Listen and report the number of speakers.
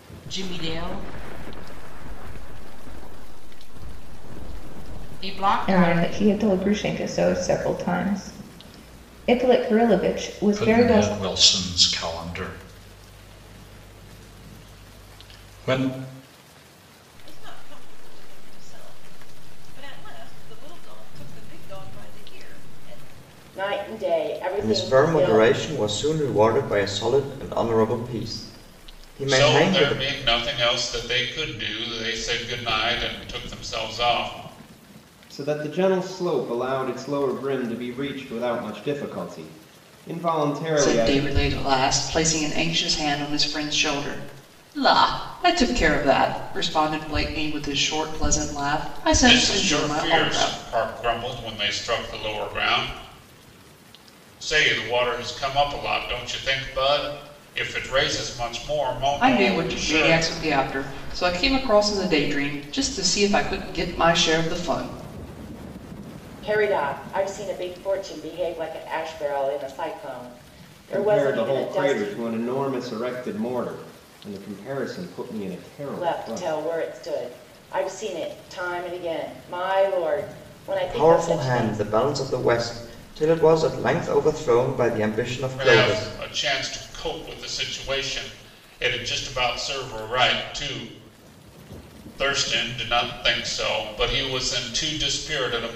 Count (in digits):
9